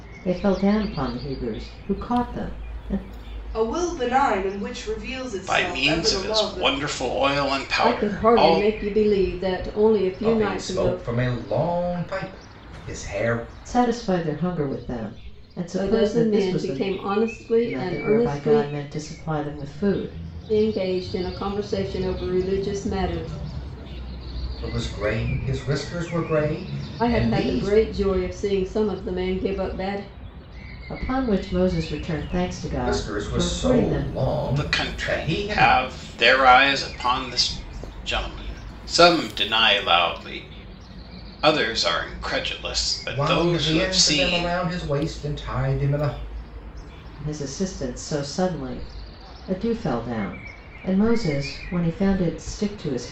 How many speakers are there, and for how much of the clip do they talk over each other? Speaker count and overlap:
five, about 19%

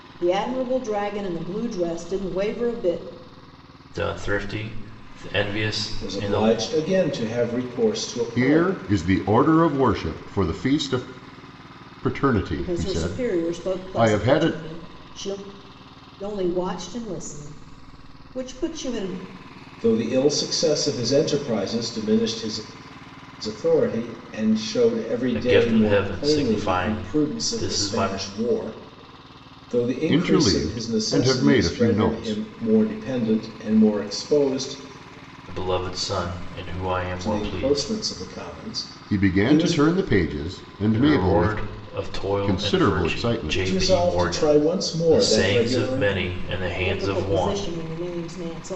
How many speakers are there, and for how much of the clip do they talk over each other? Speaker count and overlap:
four, about 31%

